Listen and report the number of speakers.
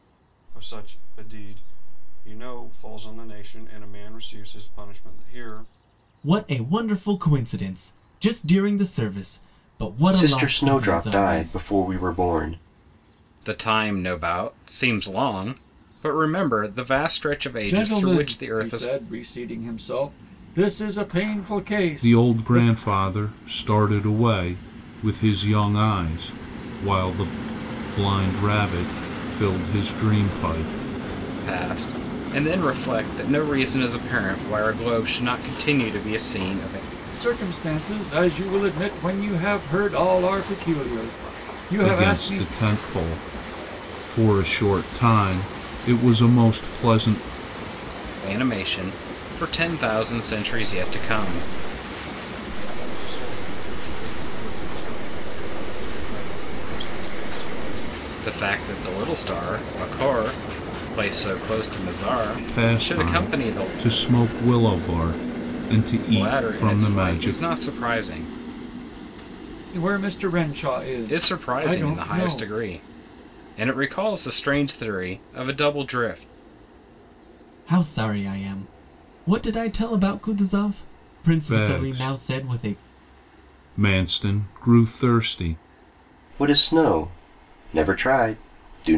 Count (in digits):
6